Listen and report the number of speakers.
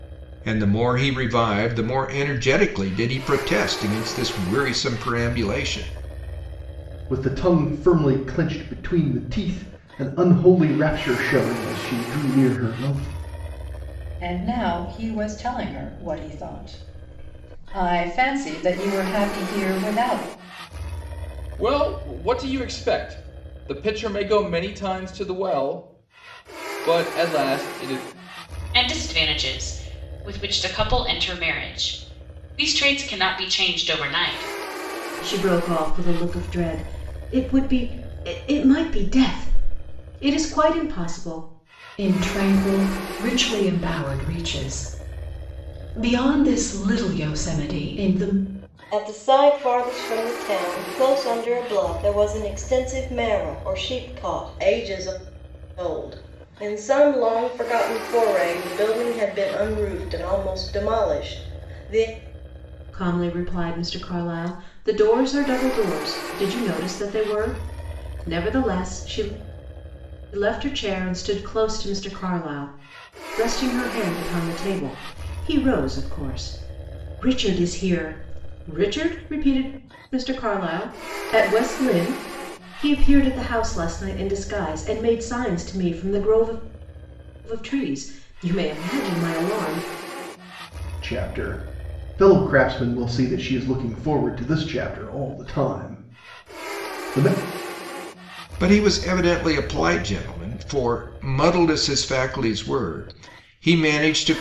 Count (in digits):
8